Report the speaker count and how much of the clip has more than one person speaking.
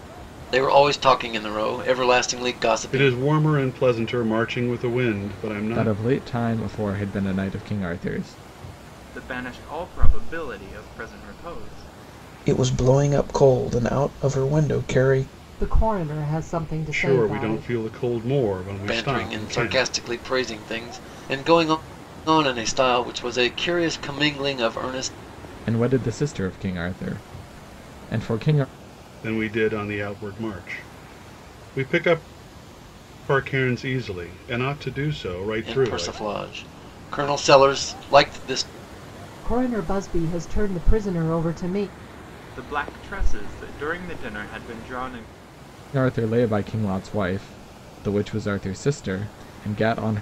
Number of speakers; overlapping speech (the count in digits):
6, about 6%